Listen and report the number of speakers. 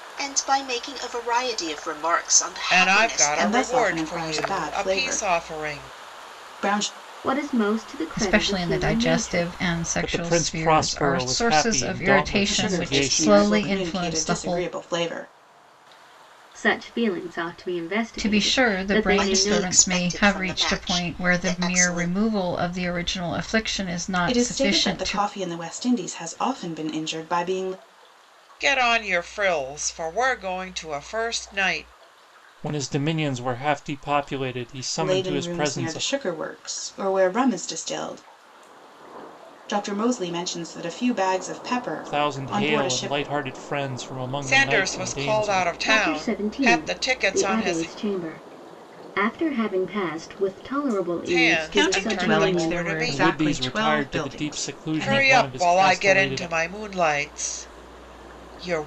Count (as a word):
six